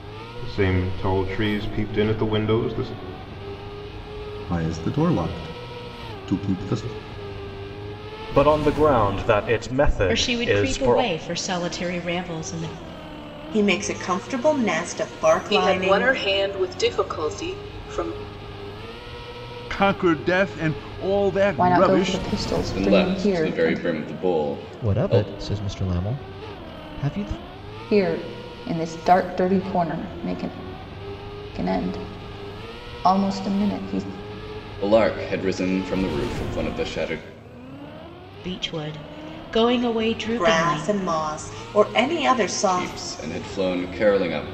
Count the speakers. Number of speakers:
10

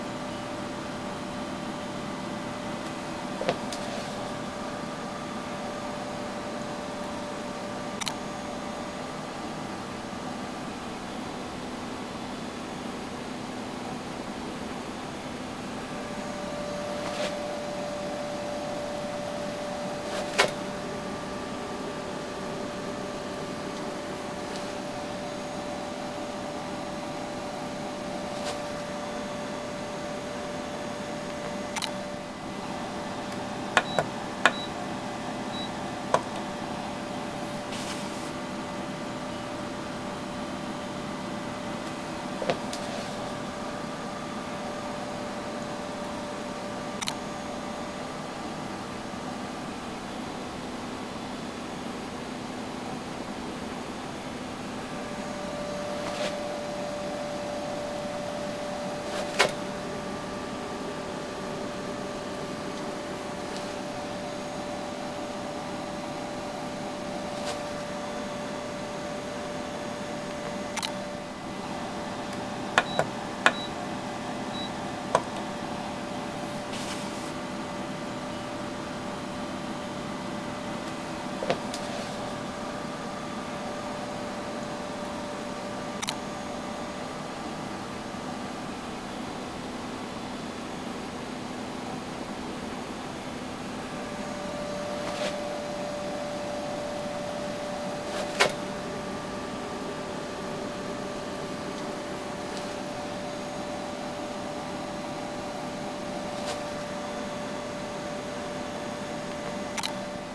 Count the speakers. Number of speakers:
0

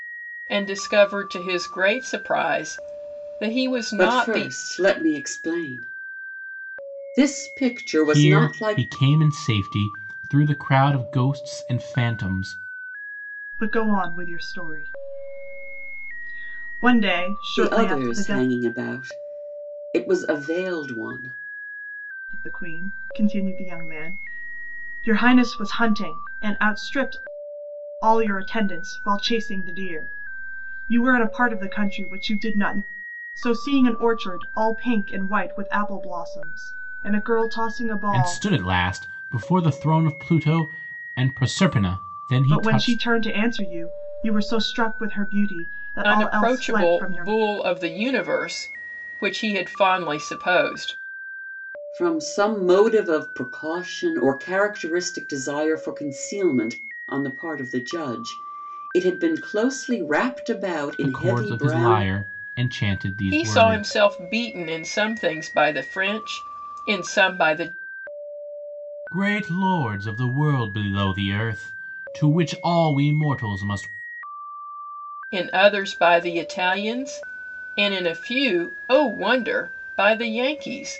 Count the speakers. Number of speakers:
4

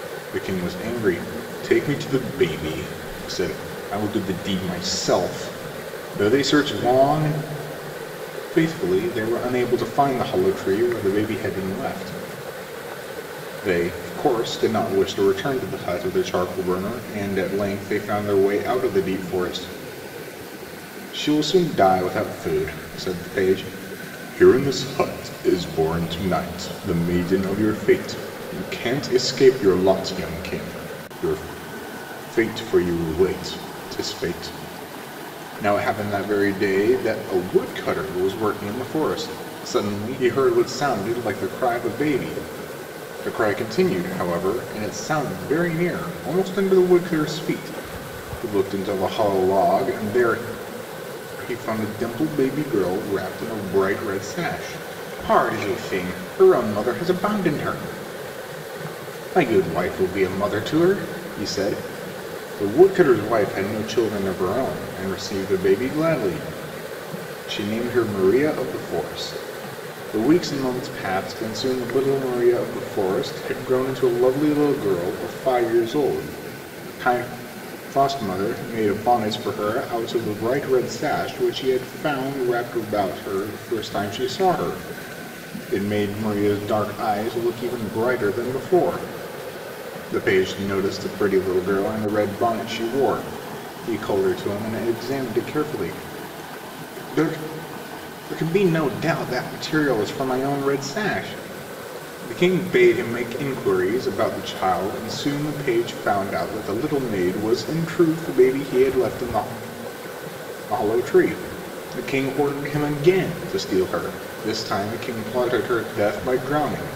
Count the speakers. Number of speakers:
1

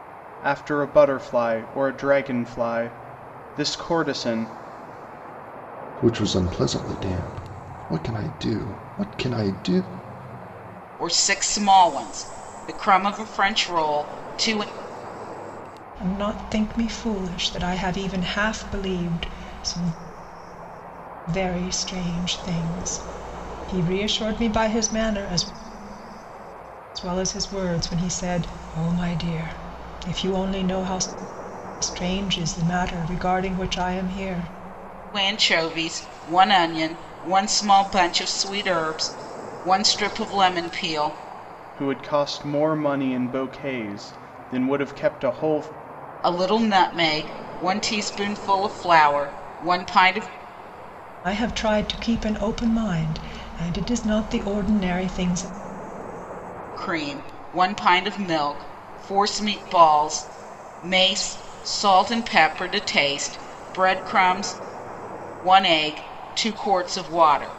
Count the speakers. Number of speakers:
4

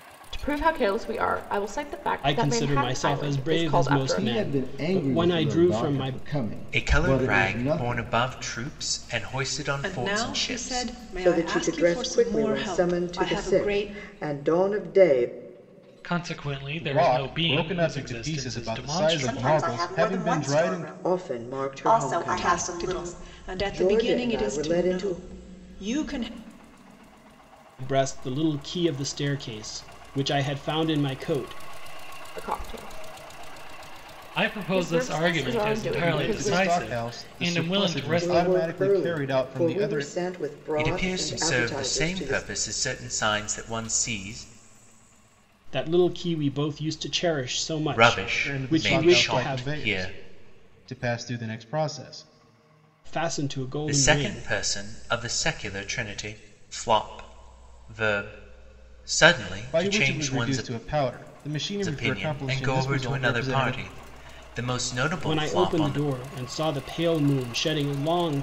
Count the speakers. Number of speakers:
9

